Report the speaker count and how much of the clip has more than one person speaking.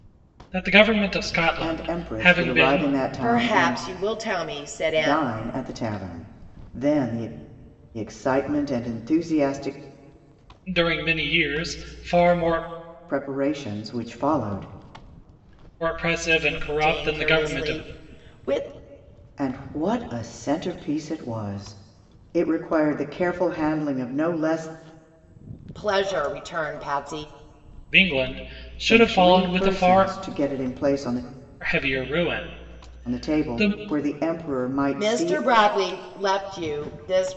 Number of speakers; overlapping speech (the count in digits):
3, about 16%